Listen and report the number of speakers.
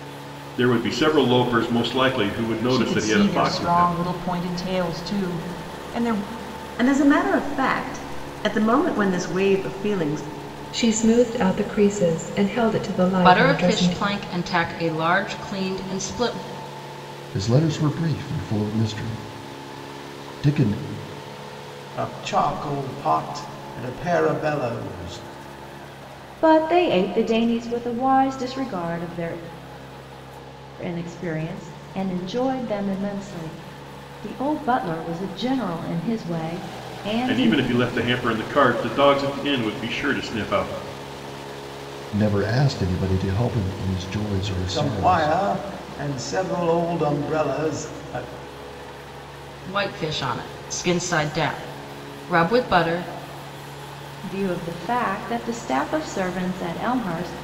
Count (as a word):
eight